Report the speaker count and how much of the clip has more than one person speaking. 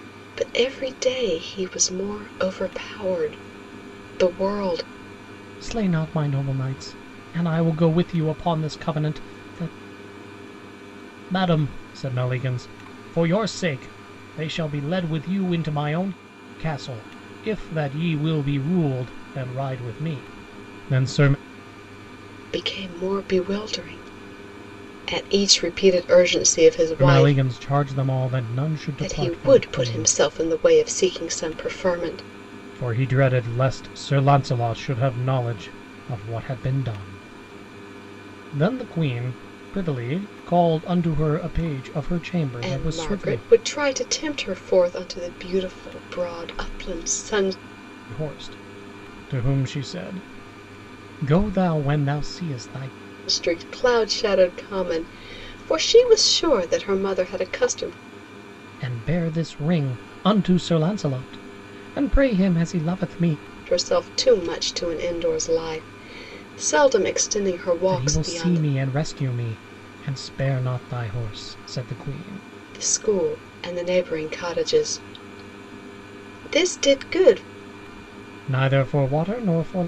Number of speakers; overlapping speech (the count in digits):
2, about 4%